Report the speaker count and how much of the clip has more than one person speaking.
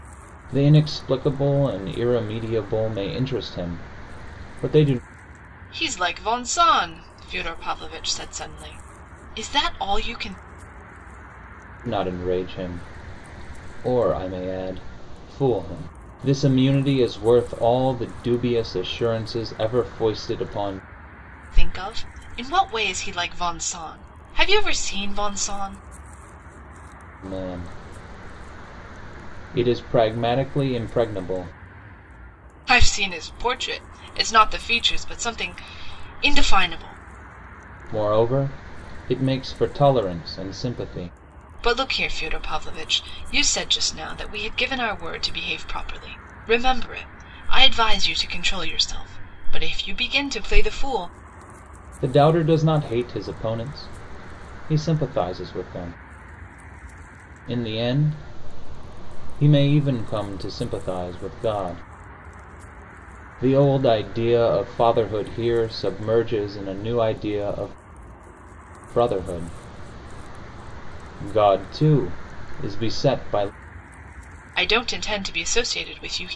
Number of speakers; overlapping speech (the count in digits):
2, no overlap